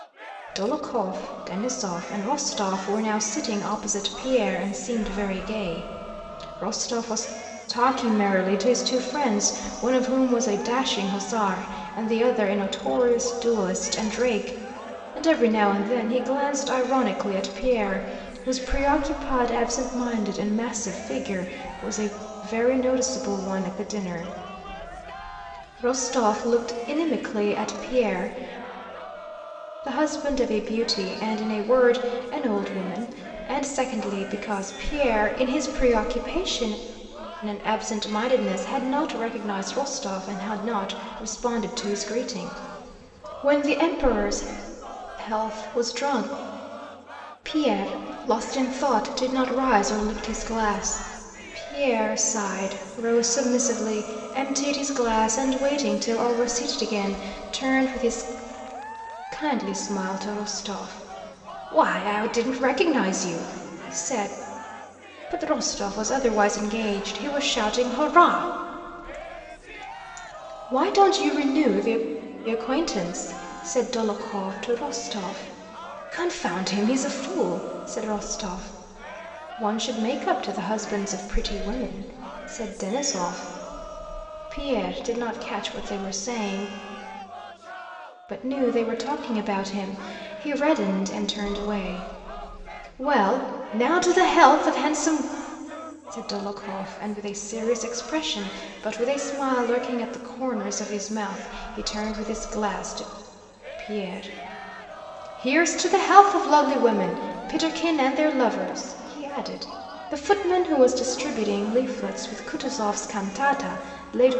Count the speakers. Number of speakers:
1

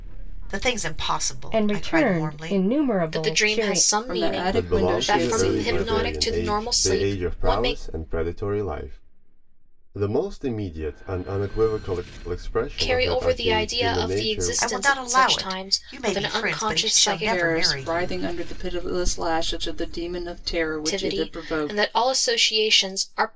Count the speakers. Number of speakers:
6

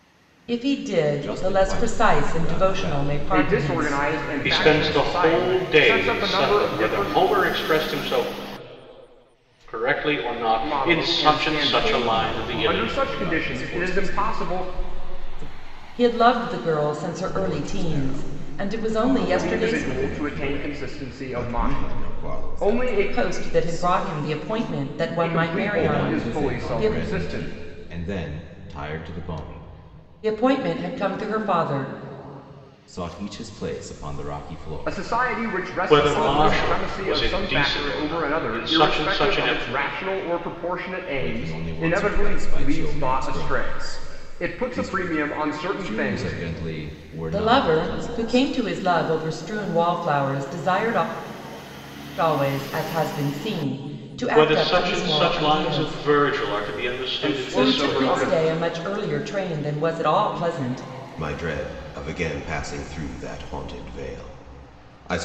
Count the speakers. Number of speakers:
4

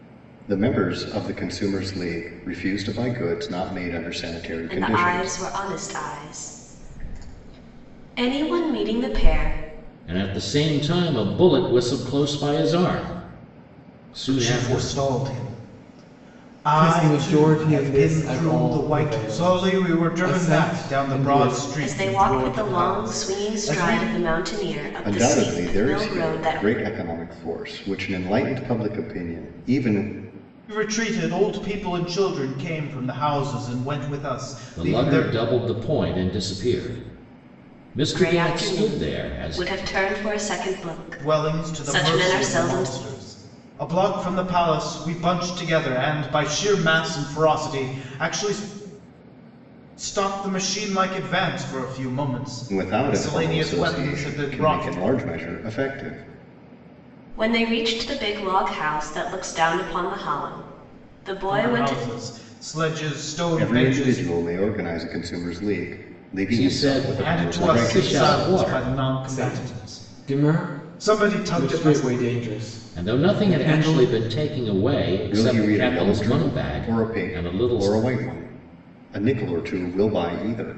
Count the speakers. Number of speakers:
5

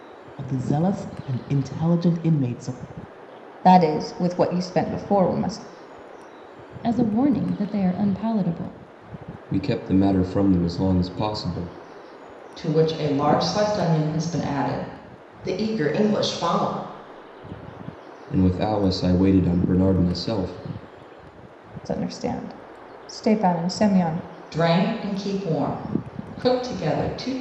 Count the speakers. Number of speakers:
6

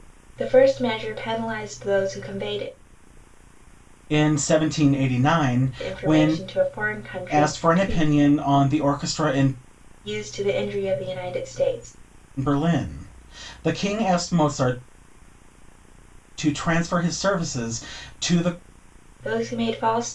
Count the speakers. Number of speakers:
2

